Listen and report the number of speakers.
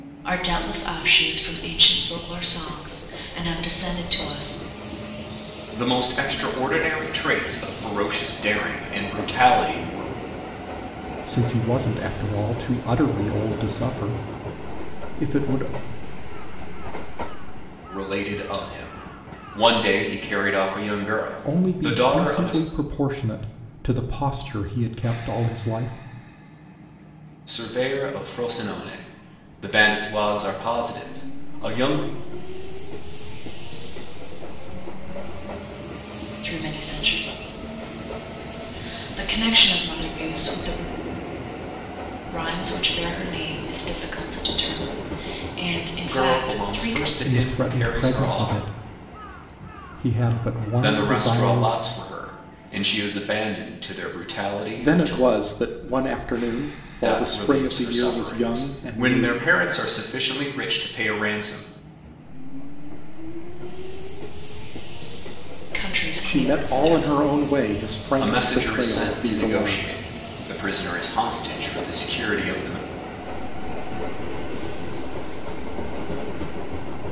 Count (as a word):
four